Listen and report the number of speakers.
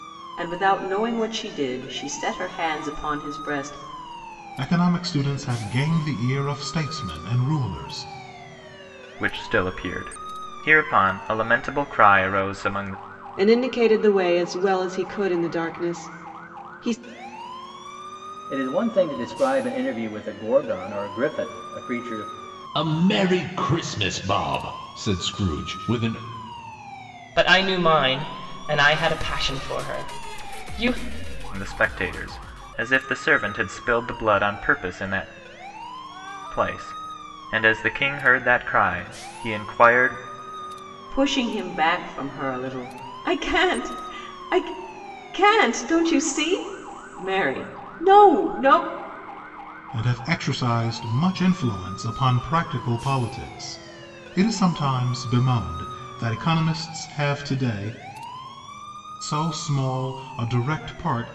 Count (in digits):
7